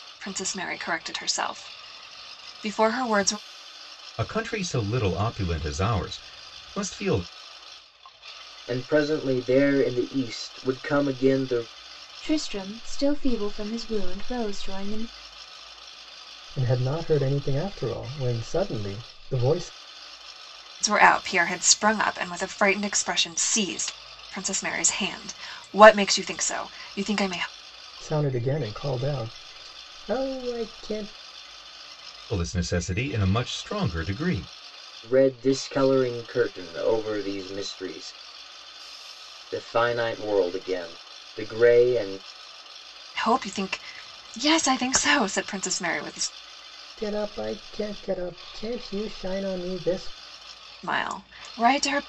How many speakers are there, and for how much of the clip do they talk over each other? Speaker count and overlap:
five, no overlap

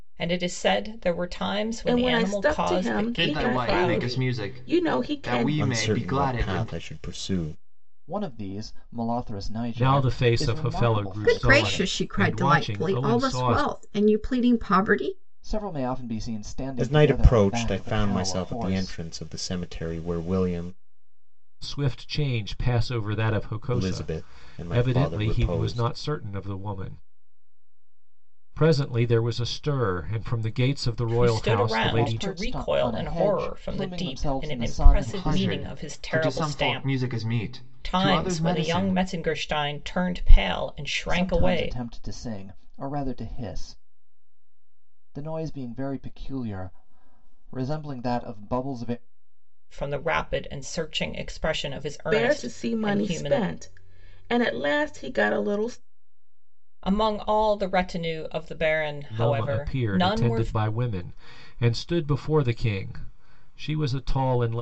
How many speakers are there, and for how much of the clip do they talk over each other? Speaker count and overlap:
seven, about 37%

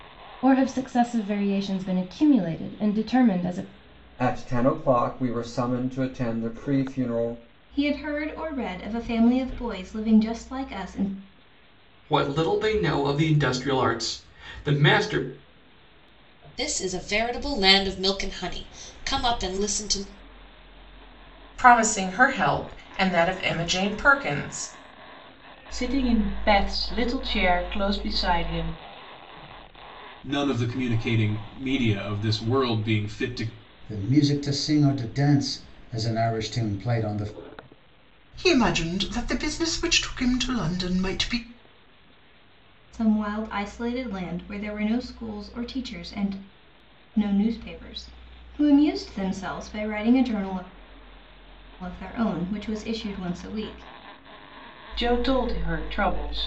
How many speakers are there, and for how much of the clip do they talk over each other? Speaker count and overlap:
ten, no overlap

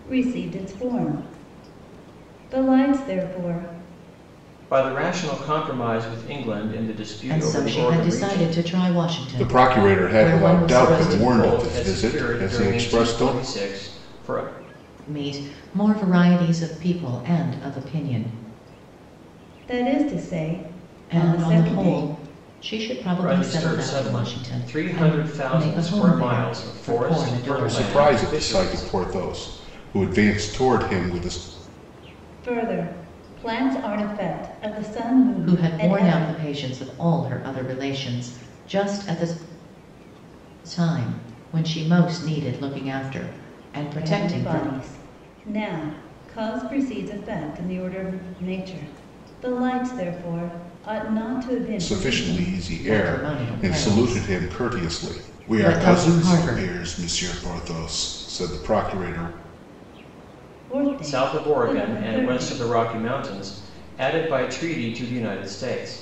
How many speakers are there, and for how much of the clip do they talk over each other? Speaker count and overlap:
four, about 29%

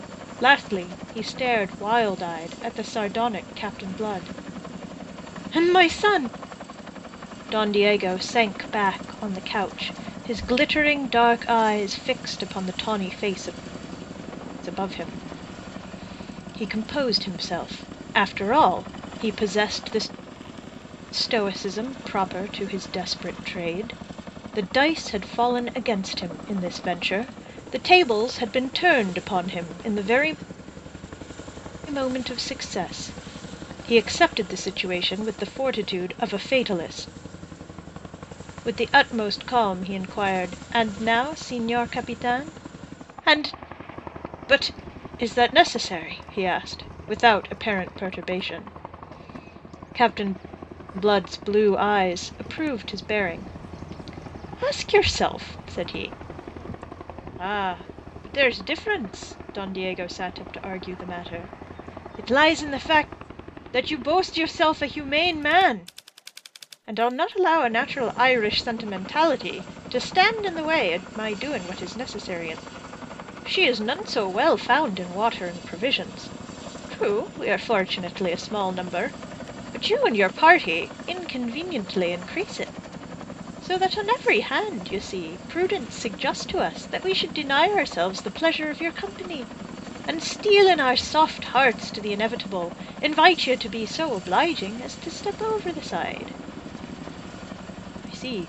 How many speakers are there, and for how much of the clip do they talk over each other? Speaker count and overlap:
one, no overlap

